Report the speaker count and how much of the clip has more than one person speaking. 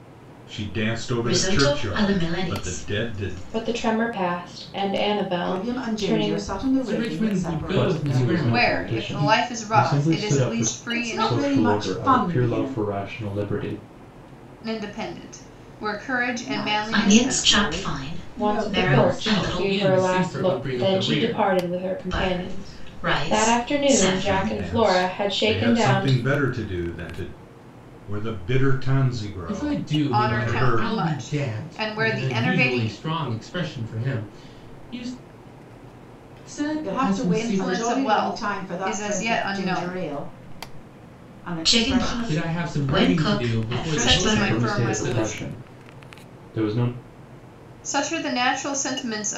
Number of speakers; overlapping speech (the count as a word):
seven, about 59%